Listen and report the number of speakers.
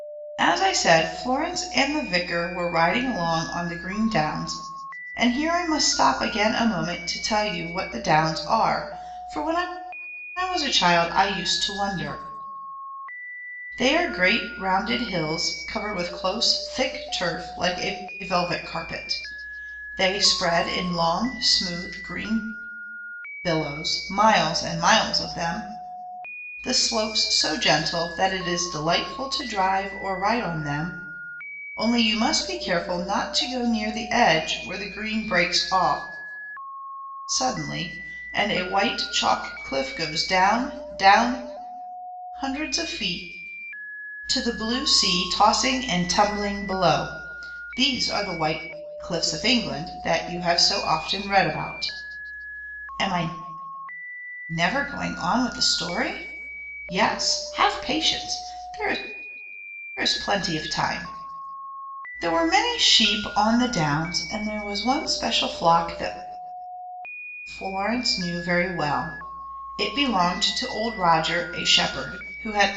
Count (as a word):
one